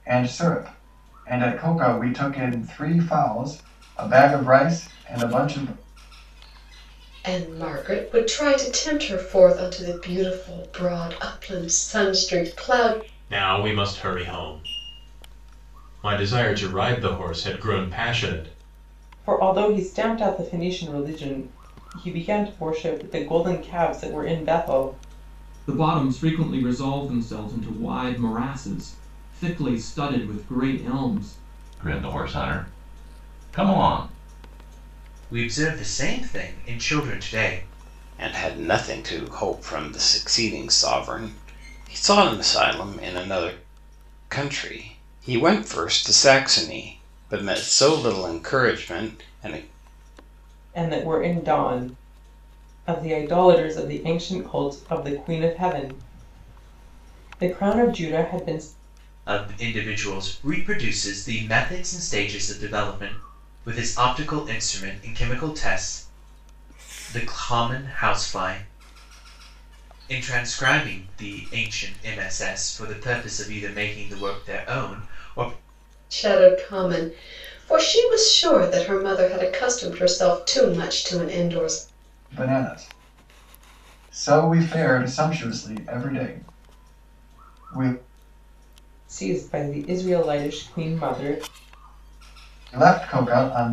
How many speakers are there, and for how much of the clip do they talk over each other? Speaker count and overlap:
eight, no overlap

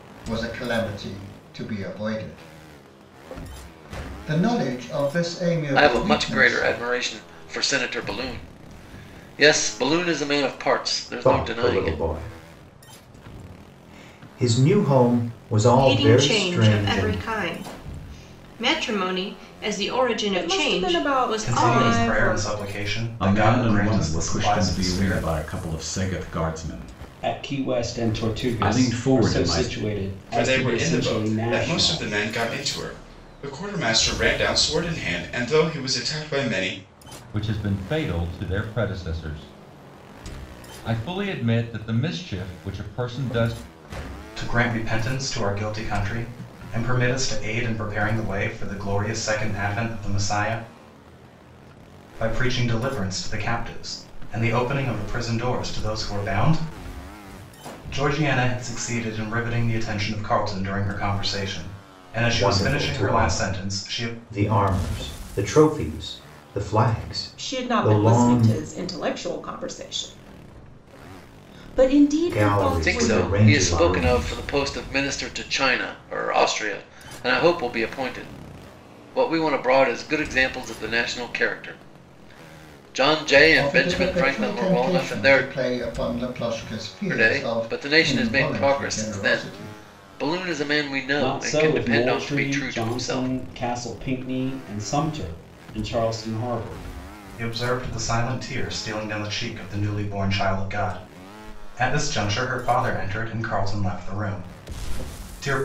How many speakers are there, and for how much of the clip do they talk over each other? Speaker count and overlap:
ten, about 23%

